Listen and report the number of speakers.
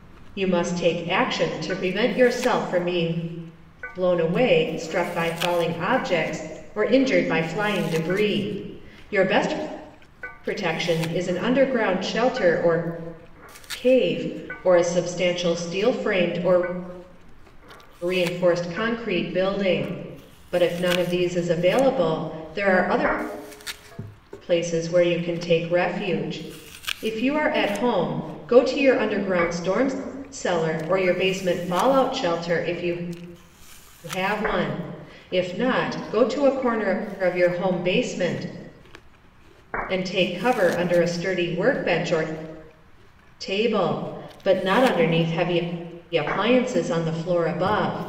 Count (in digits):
1